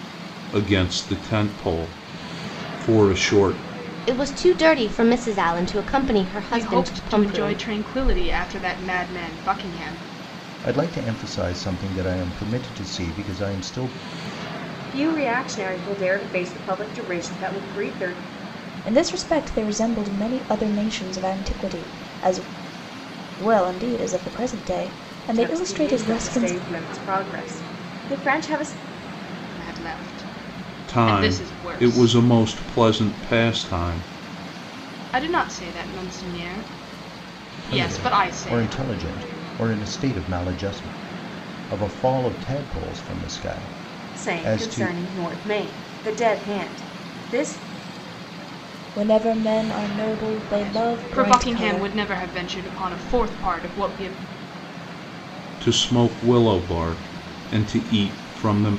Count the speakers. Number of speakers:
6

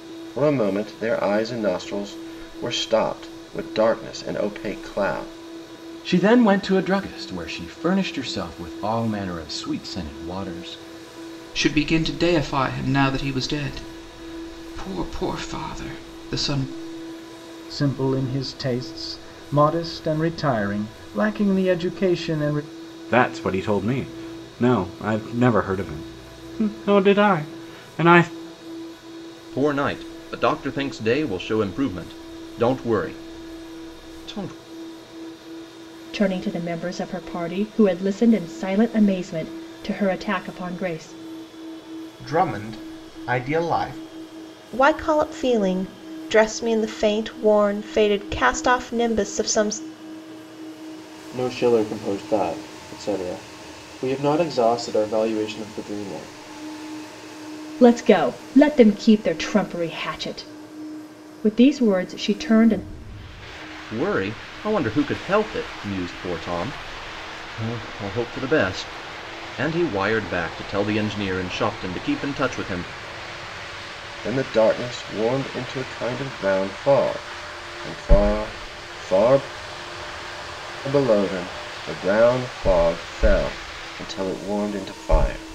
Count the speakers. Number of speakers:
10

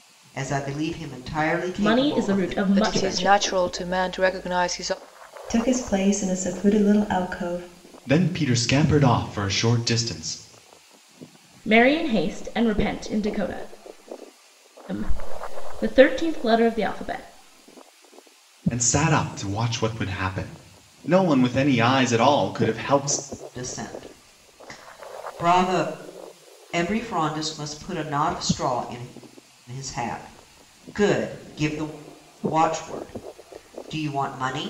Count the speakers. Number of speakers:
5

